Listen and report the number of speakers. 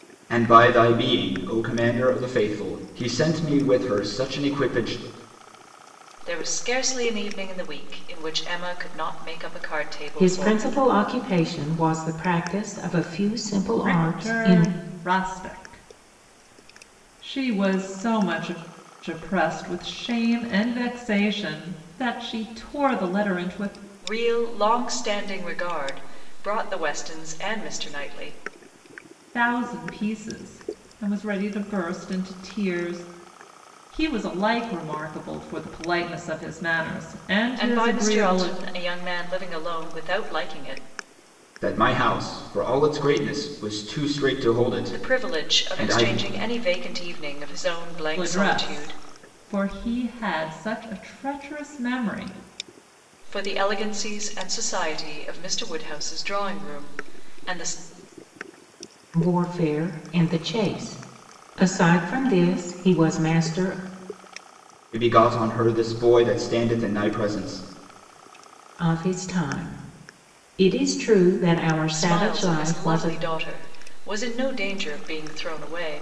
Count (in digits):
4